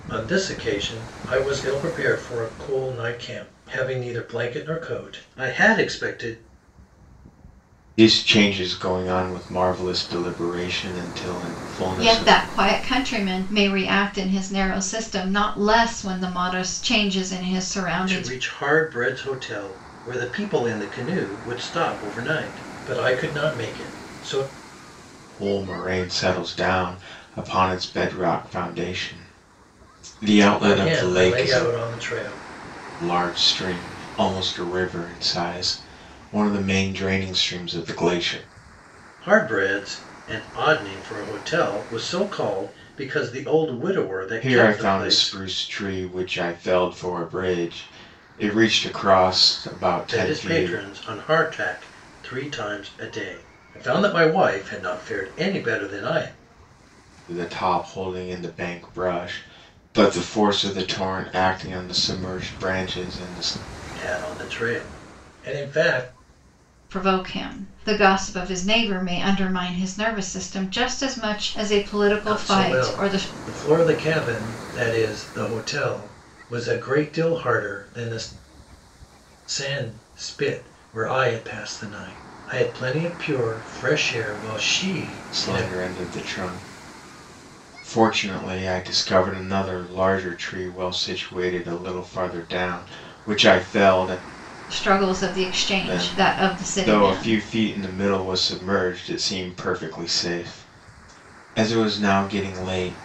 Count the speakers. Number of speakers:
3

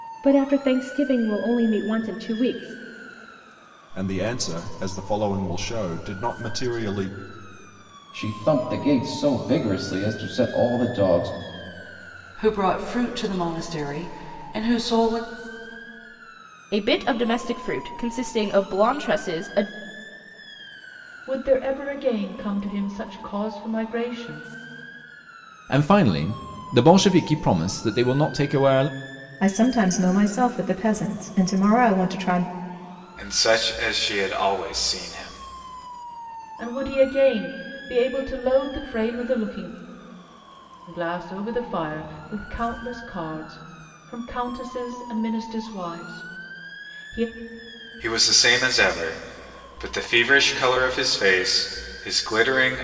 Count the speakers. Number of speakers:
9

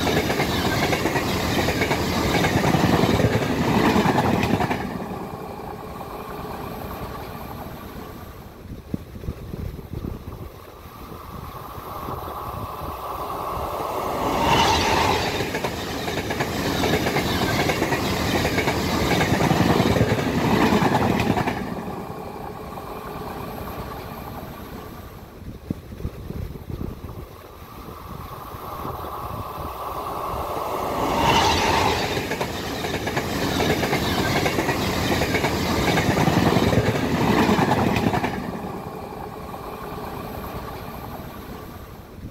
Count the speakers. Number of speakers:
0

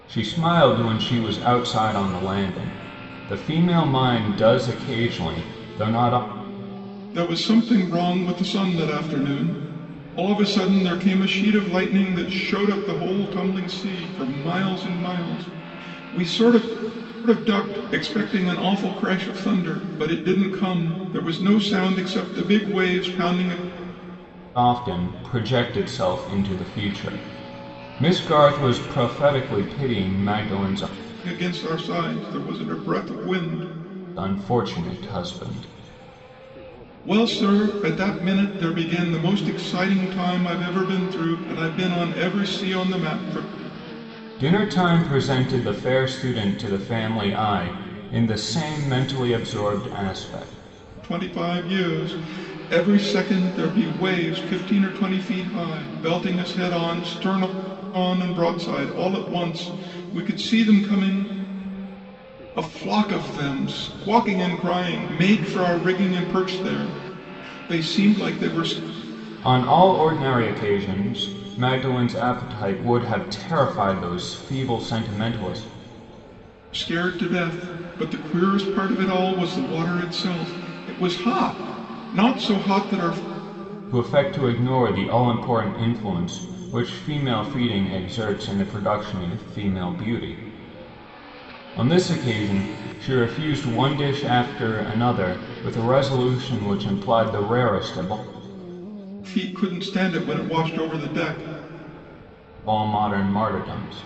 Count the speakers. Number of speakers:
2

